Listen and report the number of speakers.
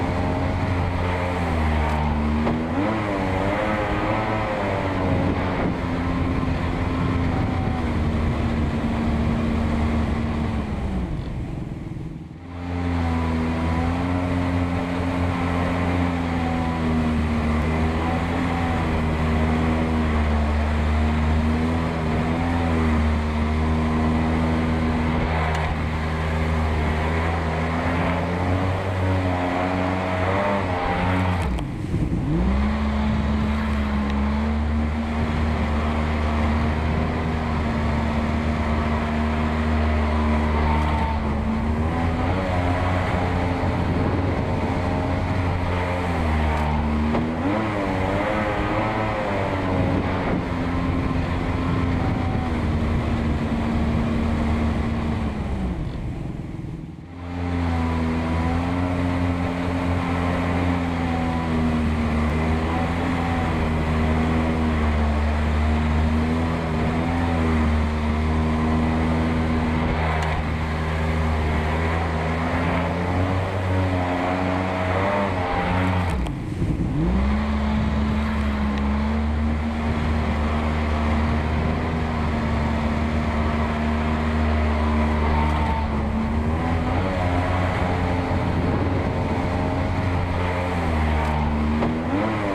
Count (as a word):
zero